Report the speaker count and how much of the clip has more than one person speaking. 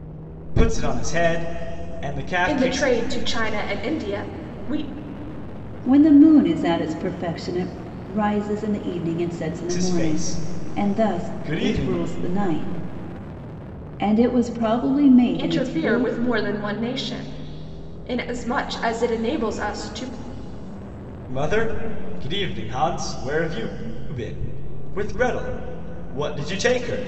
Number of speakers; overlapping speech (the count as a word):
three, about 12%